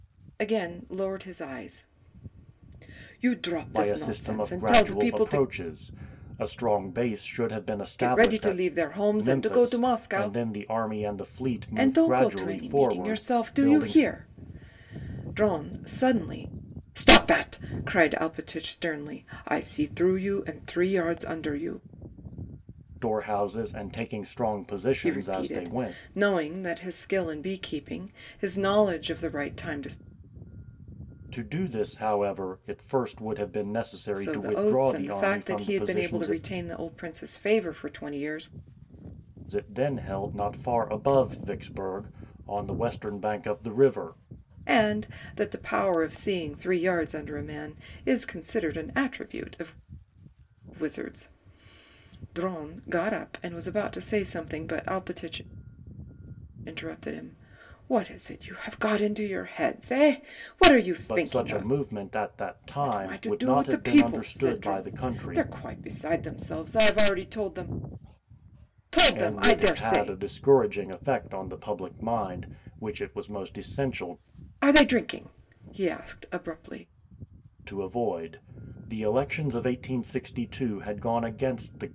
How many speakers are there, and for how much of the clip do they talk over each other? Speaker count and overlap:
two, about 17%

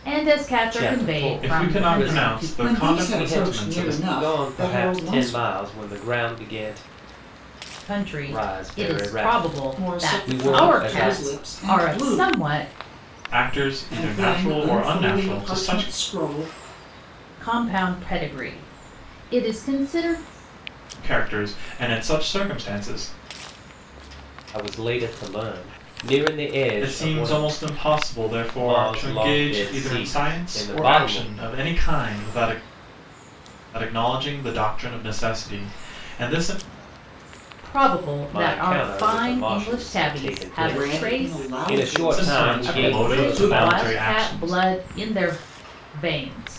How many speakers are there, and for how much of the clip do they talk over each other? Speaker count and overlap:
four, about 44%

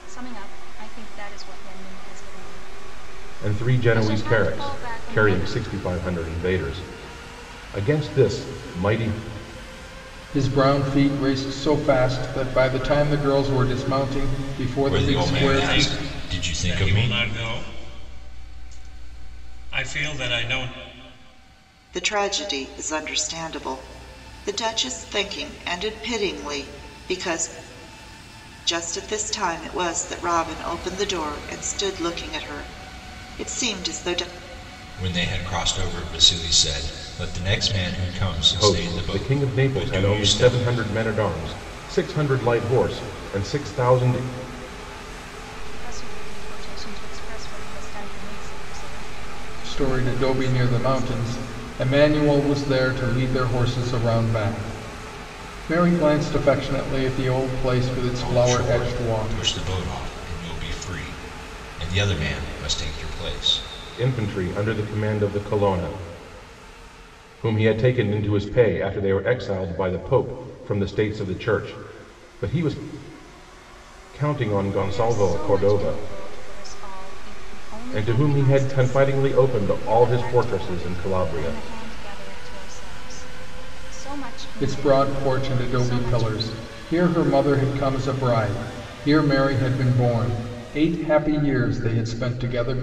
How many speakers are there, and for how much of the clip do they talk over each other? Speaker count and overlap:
six, about 17%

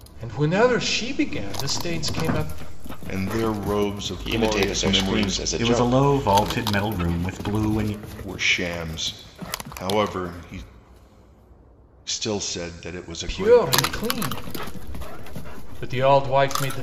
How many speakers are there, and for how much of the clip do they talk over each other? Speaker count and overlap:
four, about 19%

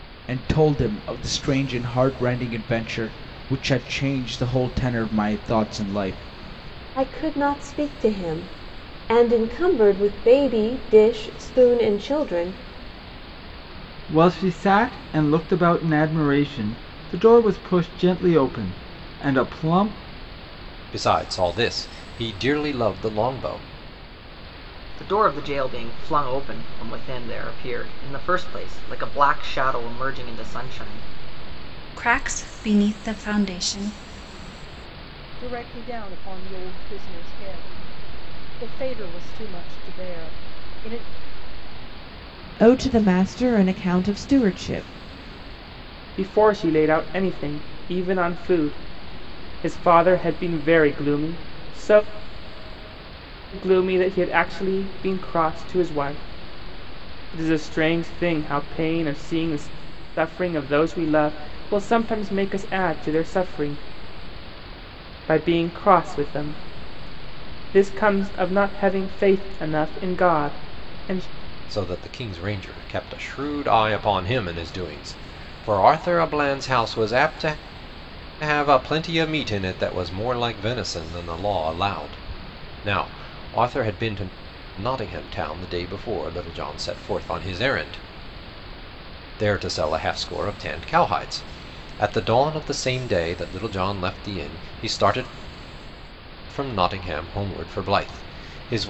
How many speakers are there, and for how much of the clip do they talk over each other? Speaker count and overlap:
nine, no overlap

